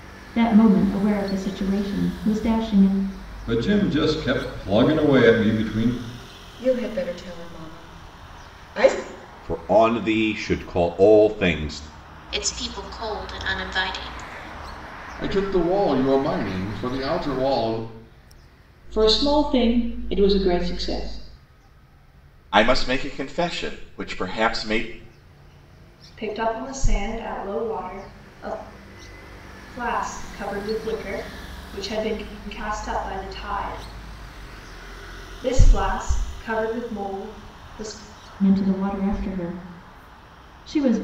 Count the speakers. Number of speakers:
9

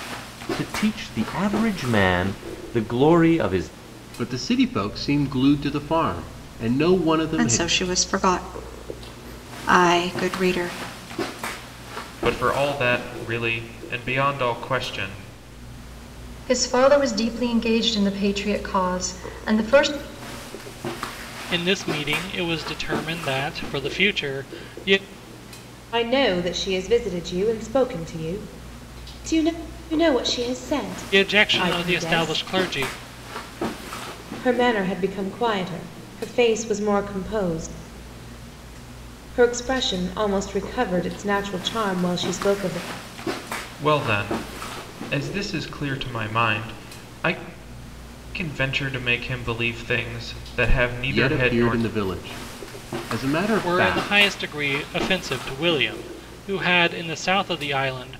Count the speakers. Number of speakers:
7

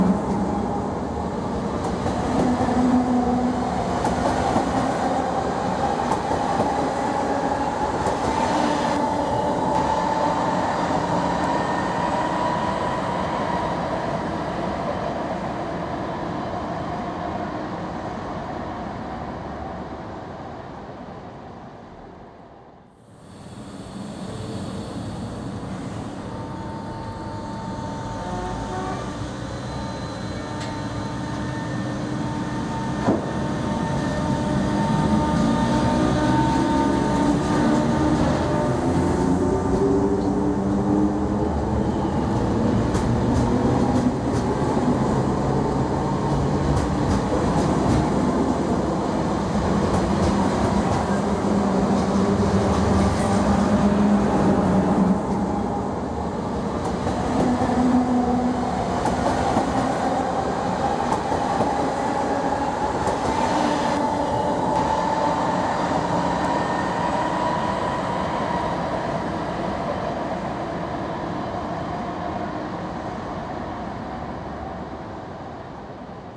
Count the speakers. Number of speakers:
0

